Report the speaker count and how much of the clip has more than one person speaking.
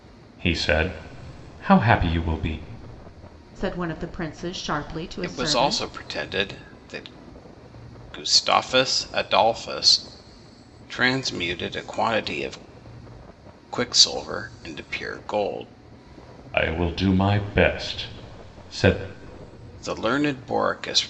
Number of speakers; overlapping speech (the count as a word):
three, about 3%